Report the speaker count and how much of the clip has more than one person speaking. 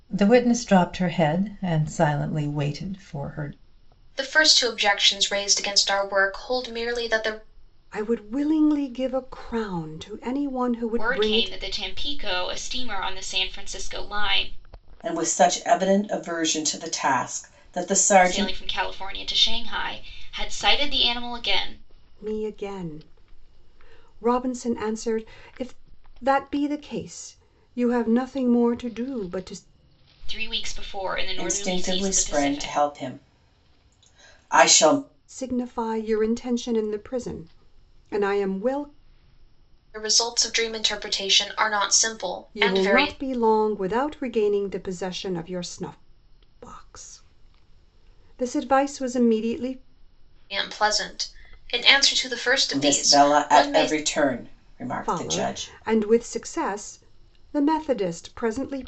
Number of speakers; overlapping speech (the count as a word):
five, about 9%